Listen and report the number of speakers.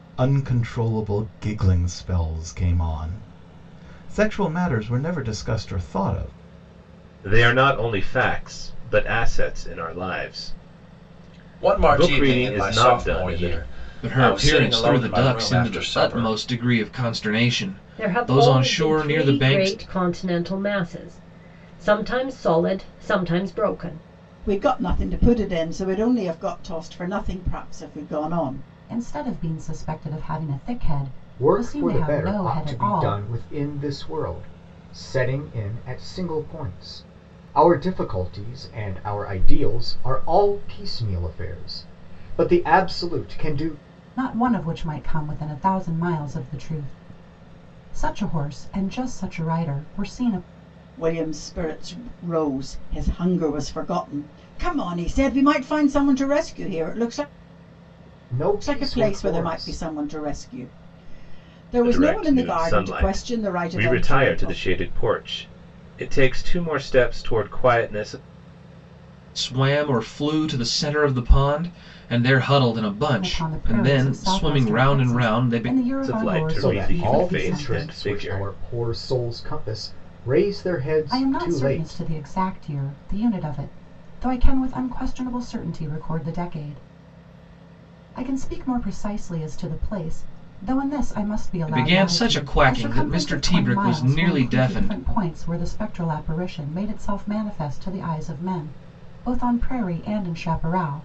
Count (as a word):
eight